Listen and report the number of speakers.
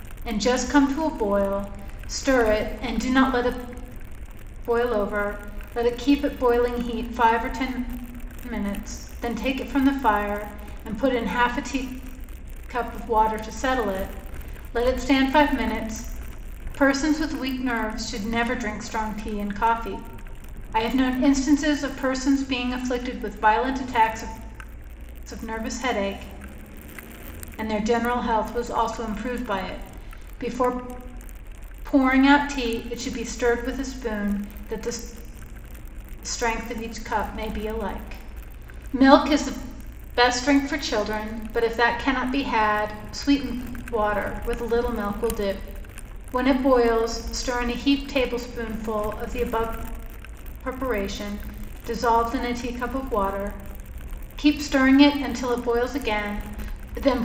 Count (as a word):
one